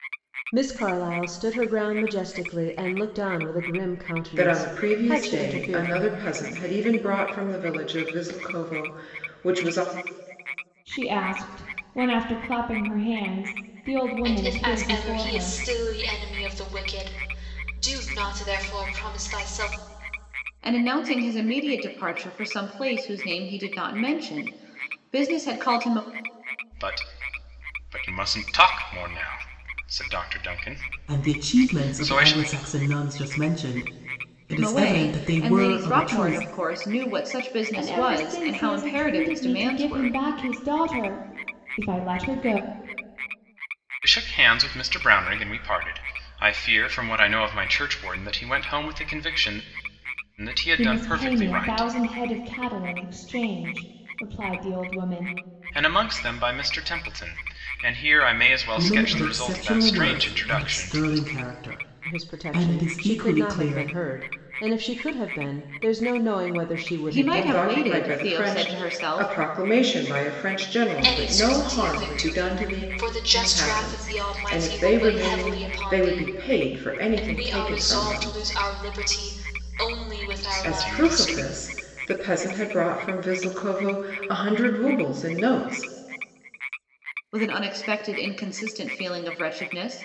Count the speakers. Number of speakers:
seven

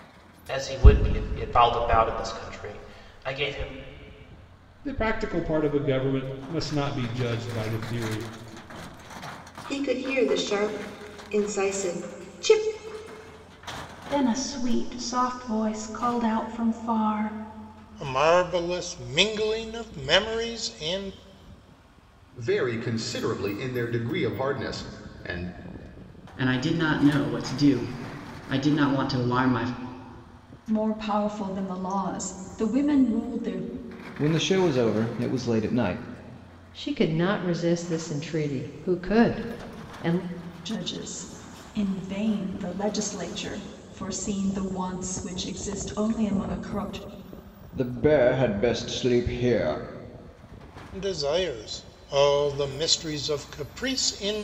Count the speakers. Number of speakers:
ten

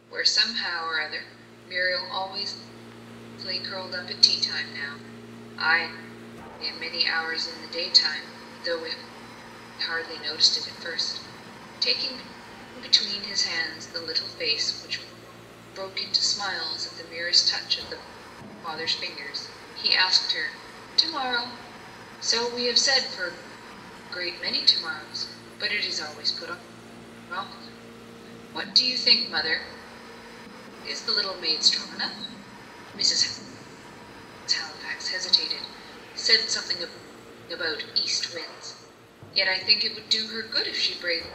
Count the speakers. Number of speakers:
one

